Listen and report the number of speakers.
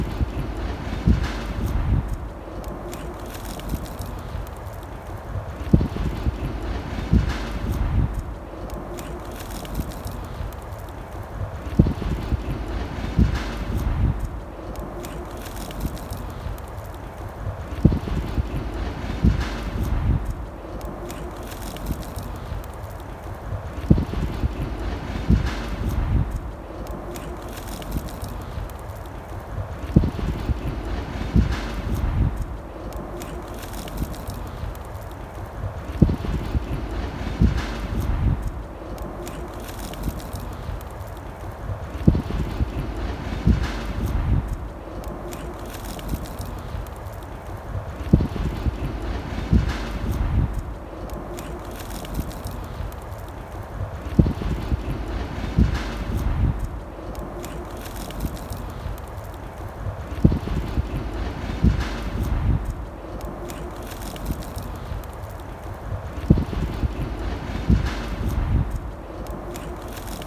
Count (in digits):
0